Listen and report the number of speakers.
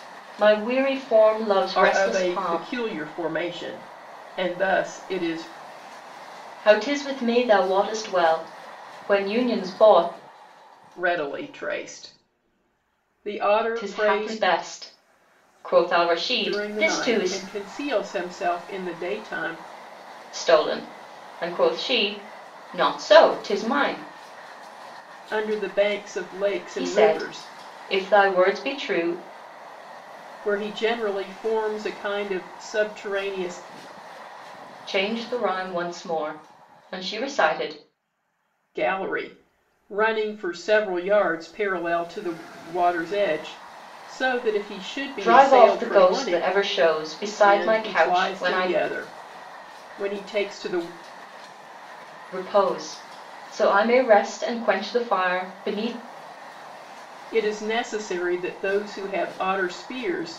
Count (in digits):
2